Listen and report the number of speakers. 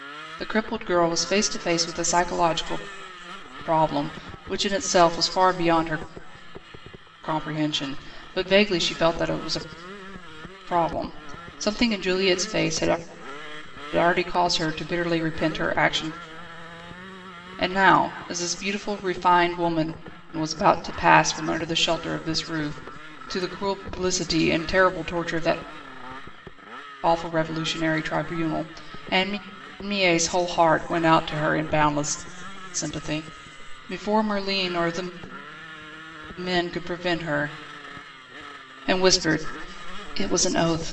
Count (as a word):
one